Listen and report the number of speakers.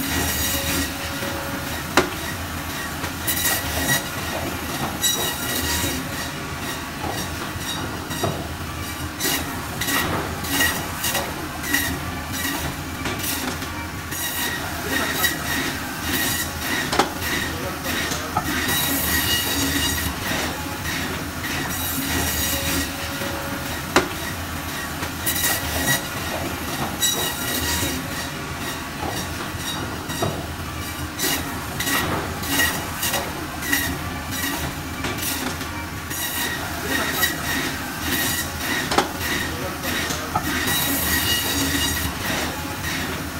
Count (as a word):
zero